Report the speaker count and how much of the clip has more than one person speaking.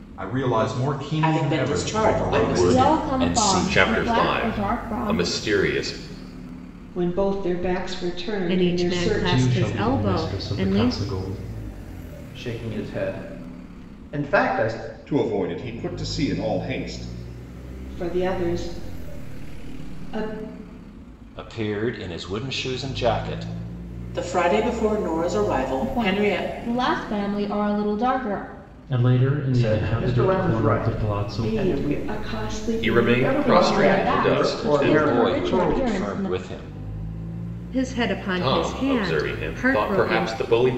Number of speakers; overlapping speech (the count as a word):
ten, about 38%